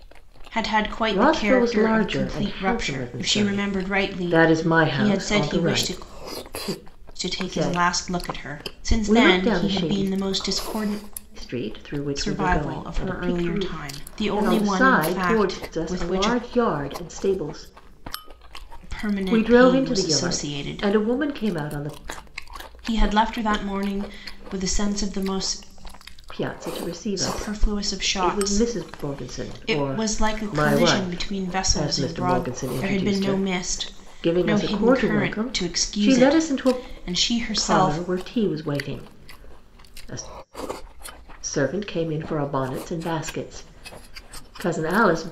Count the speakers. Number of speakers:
2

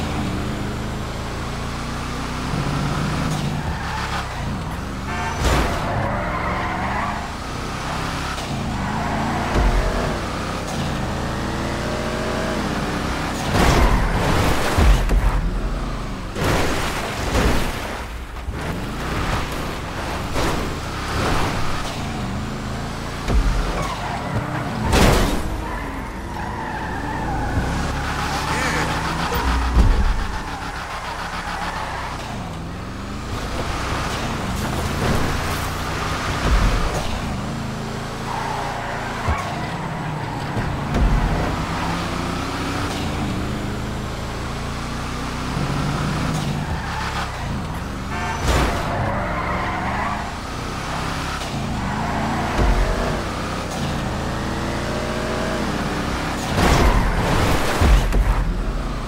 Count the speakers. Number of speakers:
0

